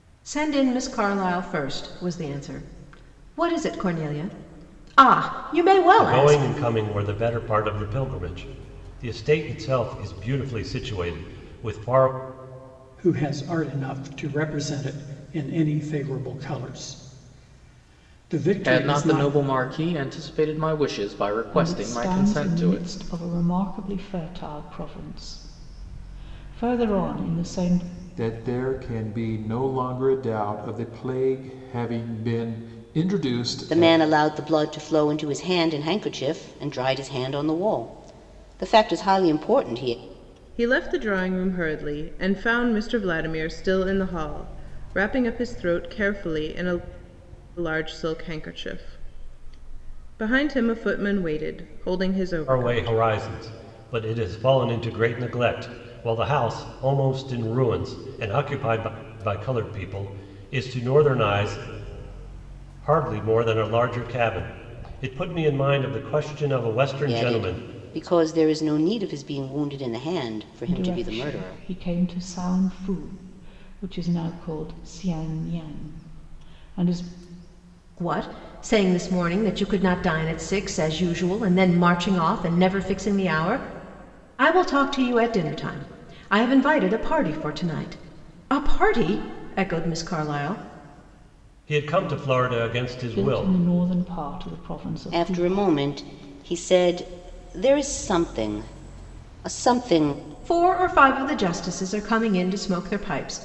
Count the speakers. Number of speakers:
8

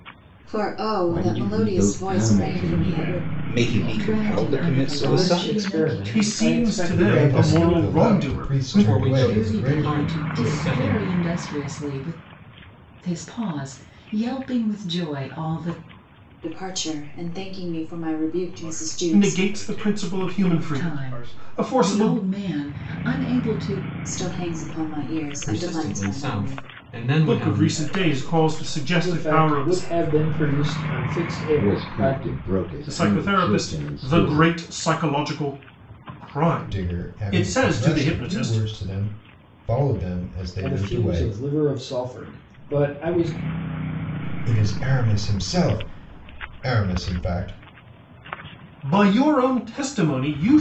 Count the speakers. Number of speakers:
9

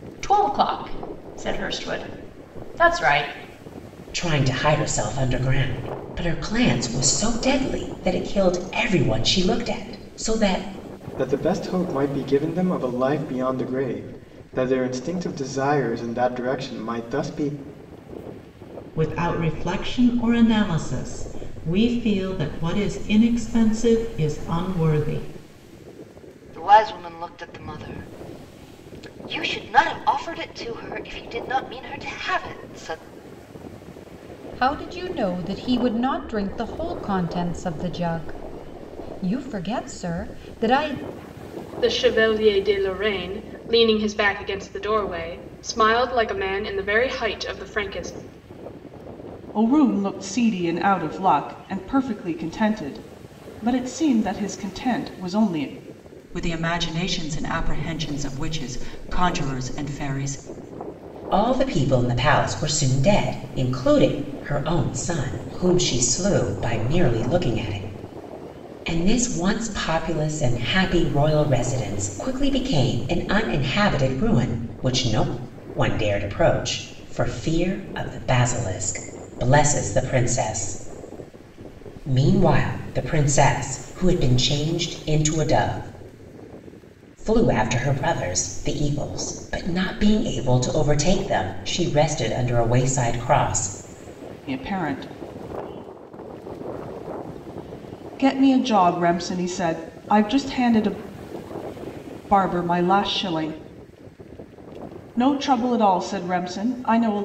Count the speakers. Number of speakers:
9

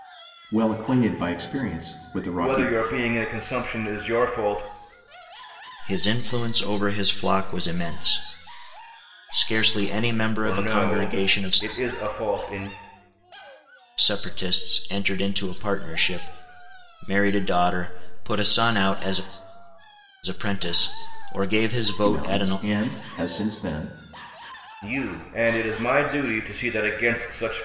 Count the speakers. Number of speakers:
3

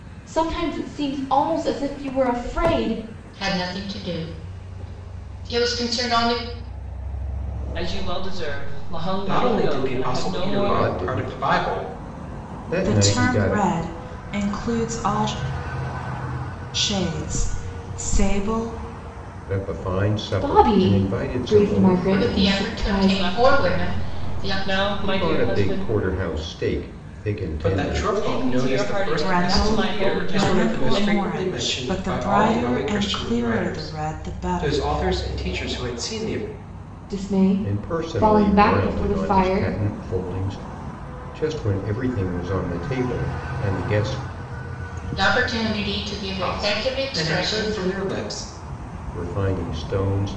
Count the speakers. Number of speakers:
6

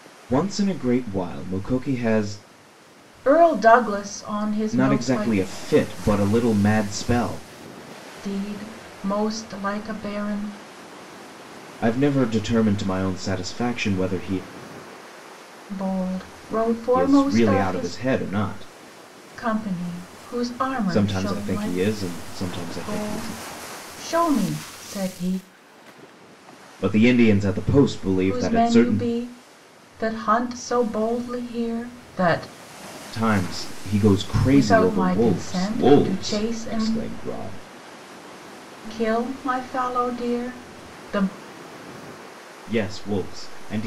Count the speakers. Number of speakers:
2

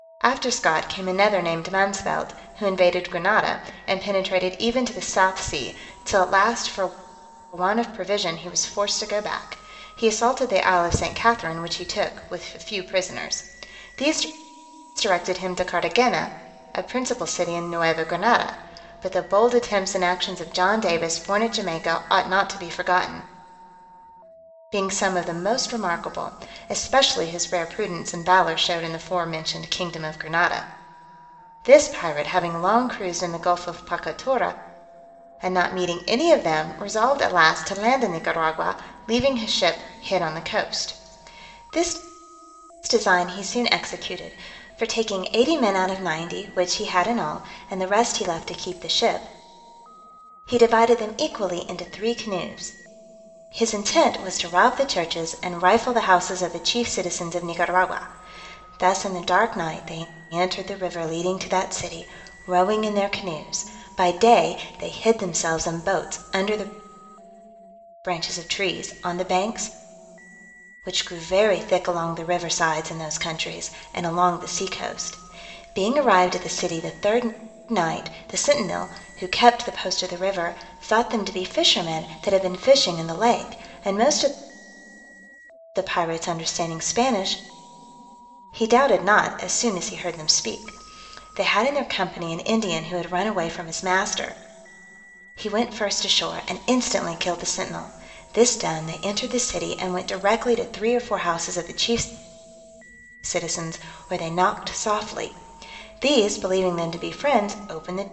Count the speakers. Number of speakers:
1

